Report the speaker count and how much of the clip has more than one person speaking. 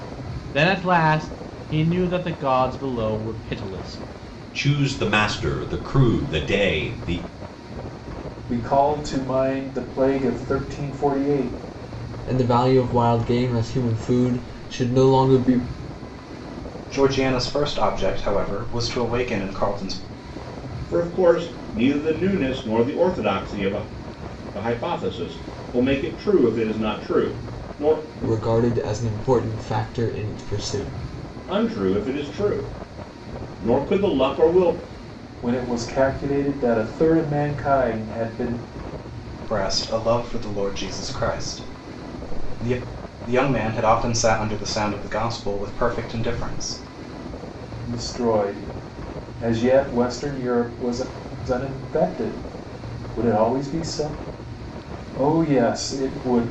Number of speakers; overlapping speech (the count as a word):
six, no overlap